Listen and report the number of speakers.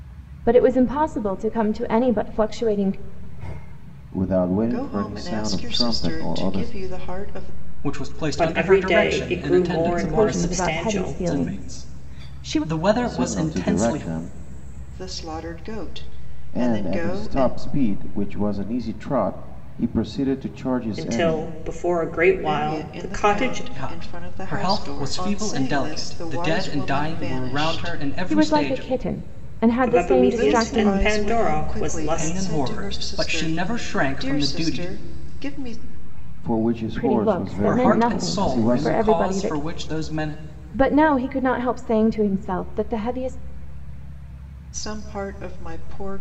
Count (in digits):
5